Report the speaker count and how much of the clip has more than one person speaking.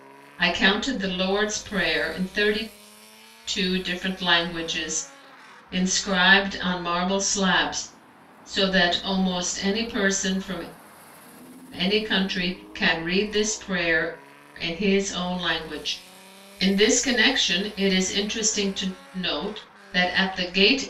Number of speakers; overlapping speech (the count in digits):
1, no overlap